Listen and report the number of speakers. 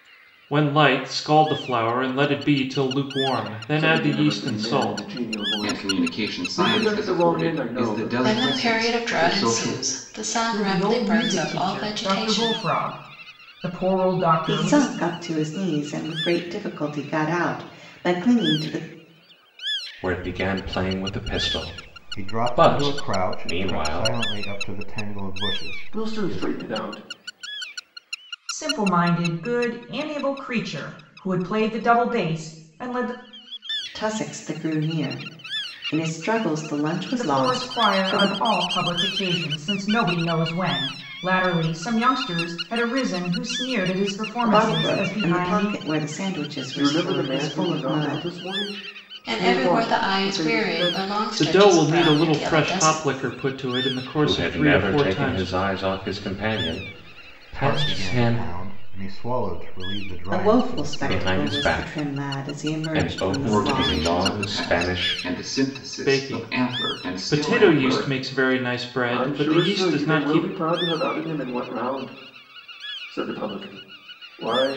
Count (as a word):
eight